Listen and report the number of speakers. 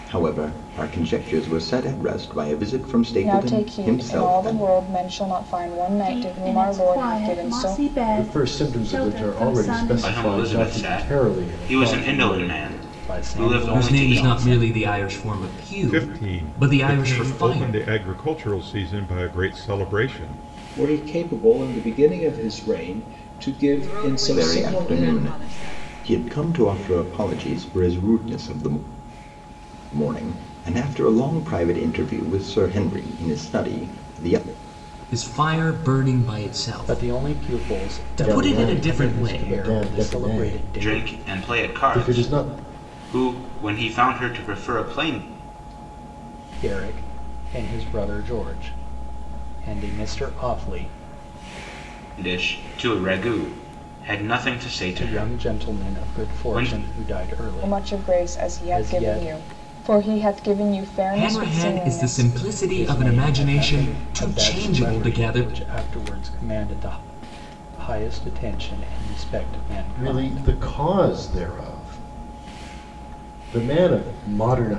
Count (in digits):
10